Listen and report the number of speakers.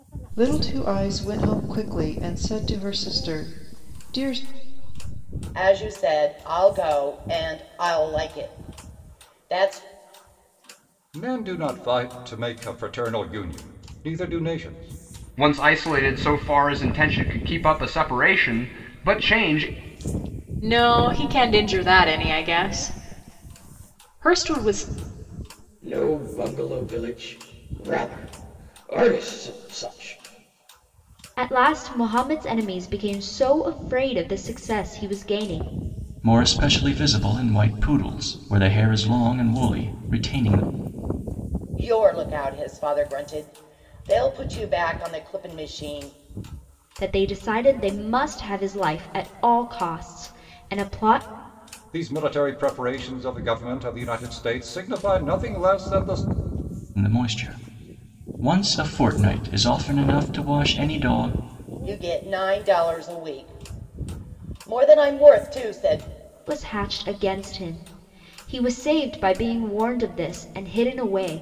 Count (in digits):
8